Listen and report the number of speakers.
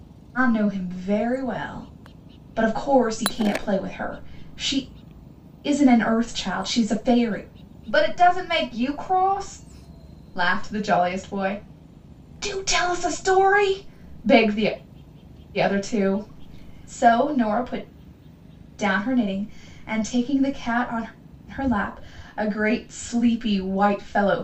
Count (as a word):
one